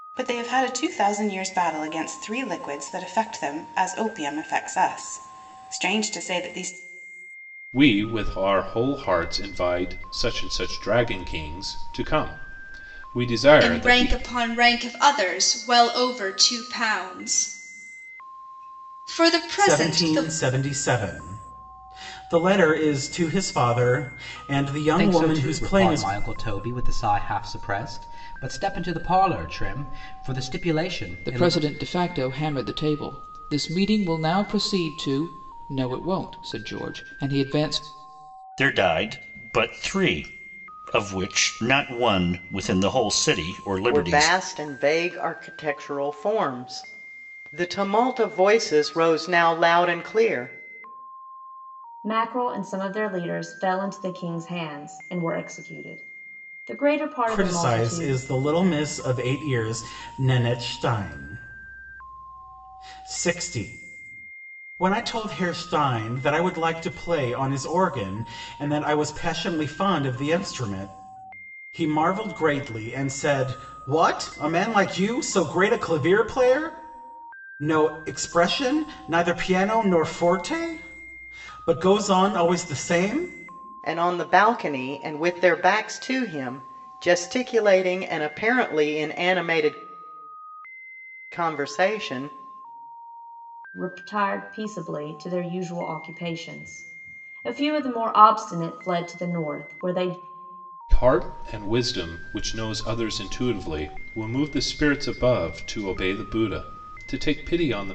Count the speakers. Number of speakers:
9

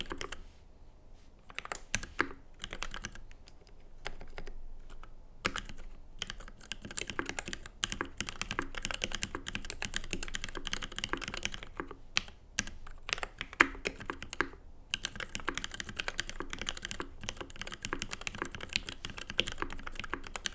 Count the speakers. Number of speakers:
0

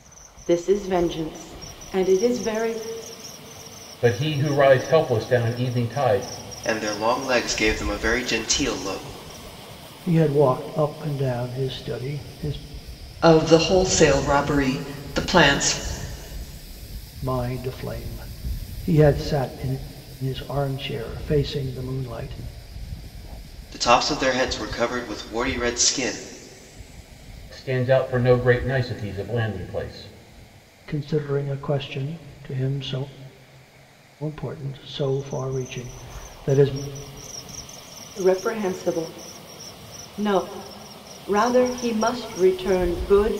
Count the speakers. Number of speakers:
5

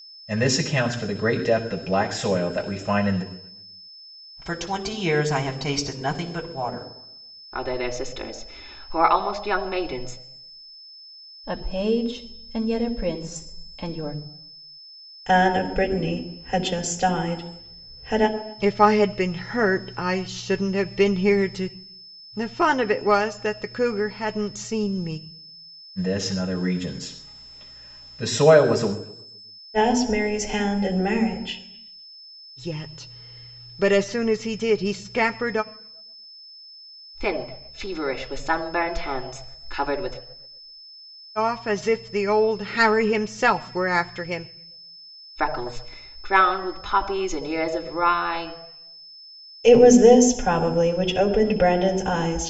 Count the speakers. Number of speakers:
6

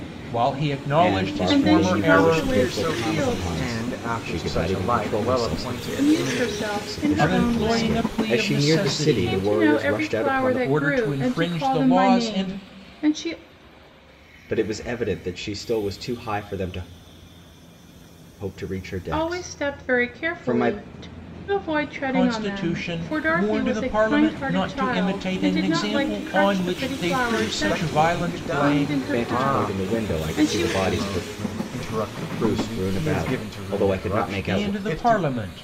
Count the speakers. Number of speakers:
4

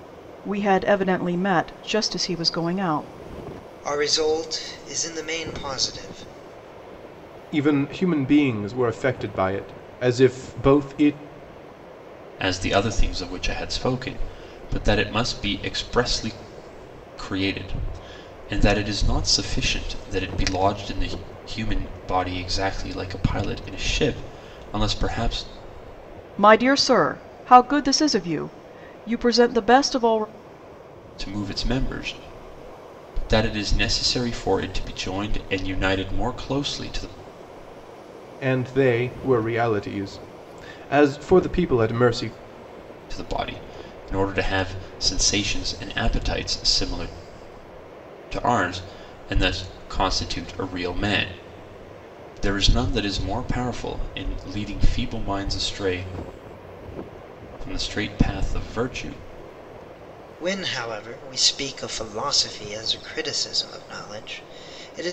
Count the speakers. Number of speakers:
4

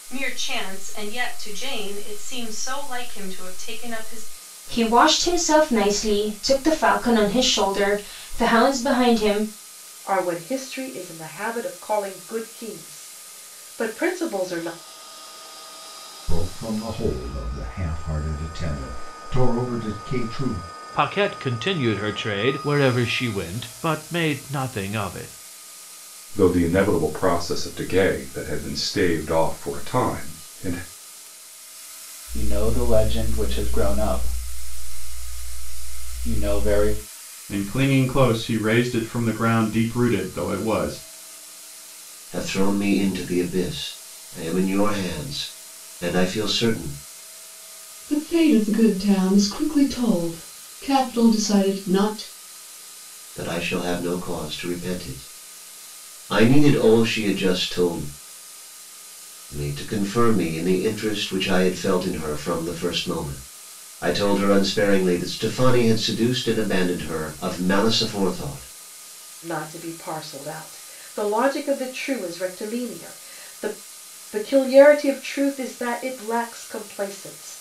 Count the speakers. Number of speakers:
10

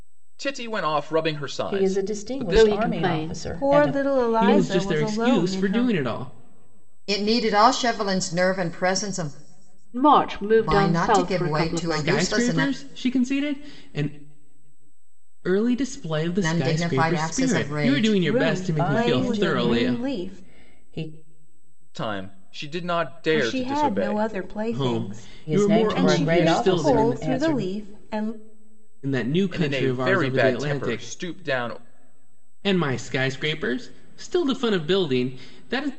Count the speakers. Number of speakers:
6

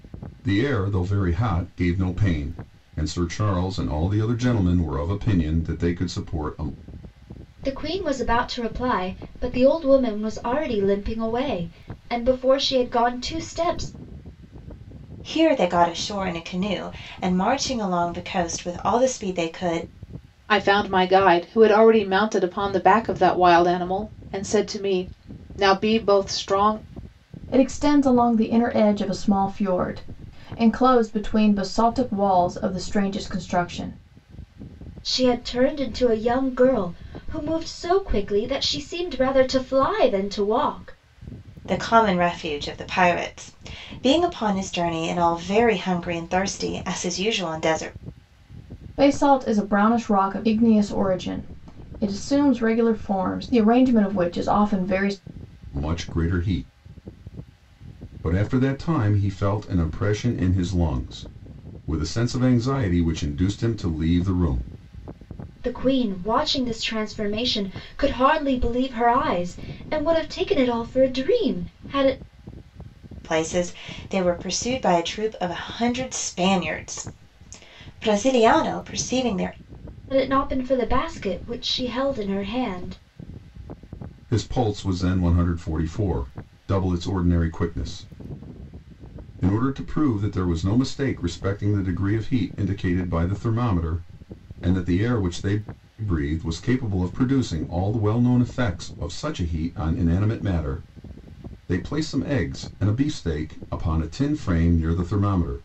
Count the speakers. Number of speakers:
5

